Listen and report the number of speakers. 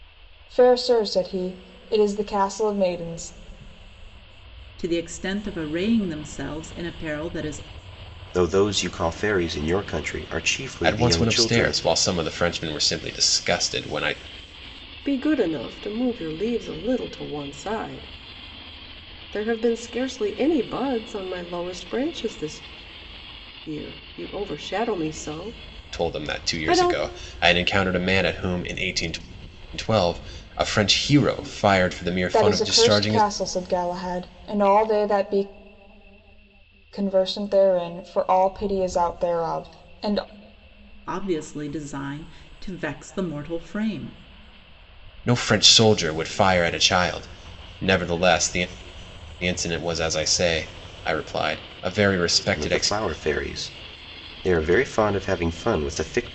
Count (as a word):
five